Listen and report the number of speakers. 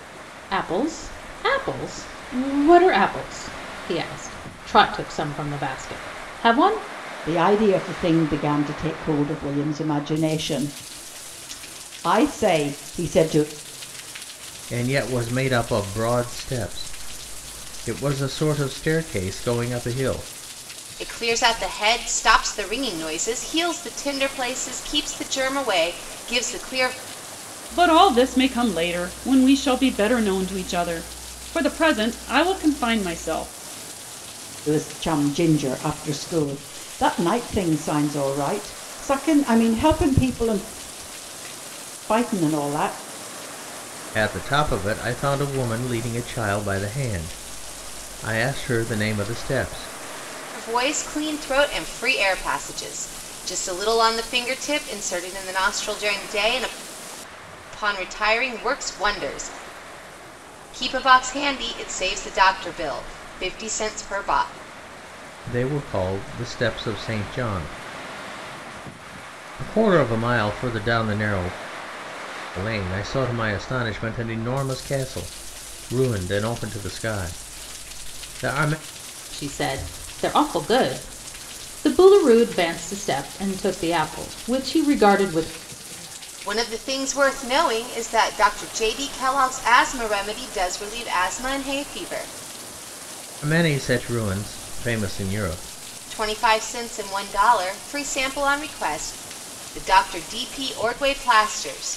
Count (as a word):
five